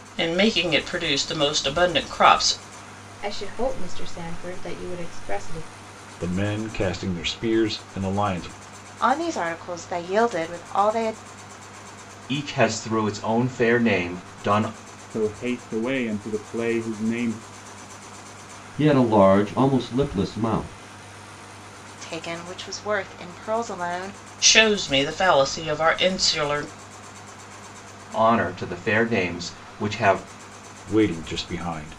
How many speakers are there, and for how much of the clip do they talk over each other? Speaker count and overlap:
7, no overlap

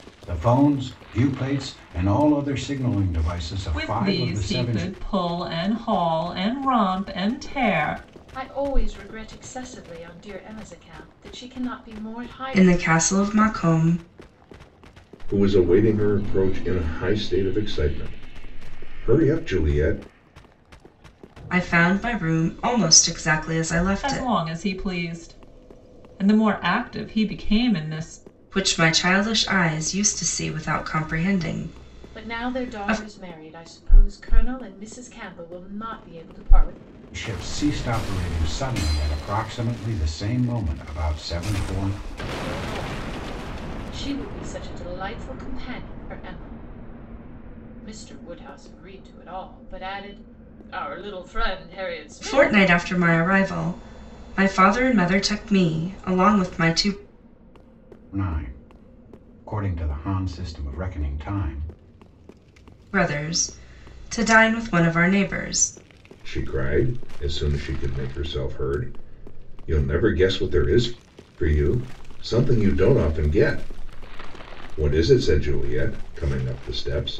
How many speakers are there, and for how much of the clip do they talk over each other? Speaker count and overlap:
5, about 4%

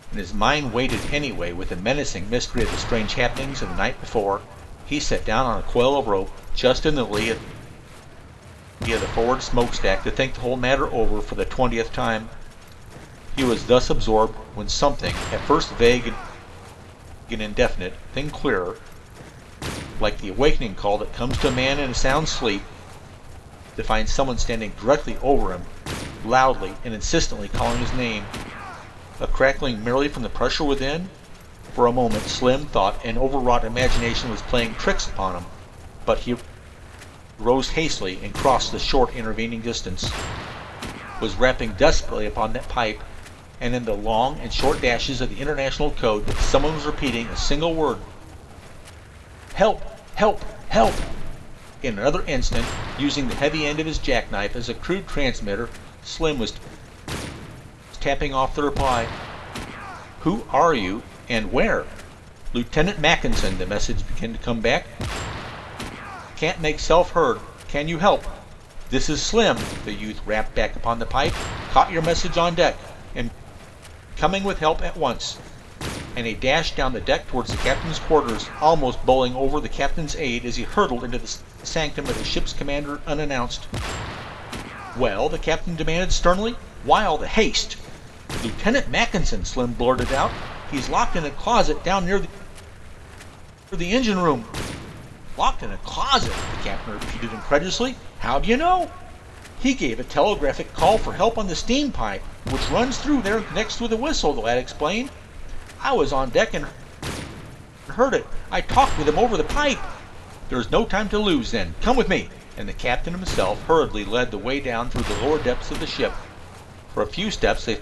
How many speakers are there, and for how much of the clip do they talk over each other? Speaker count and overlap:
1, no overlap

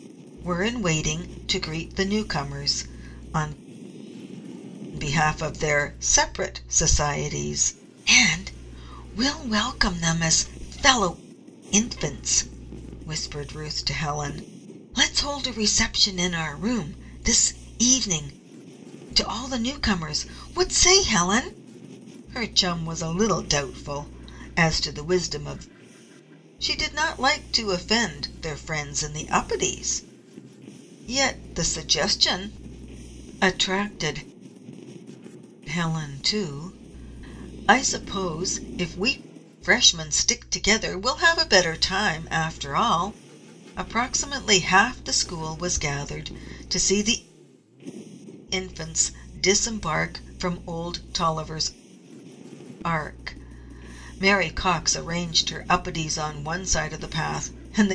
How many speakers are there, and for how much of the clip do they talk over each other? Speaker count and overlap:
1, no overlap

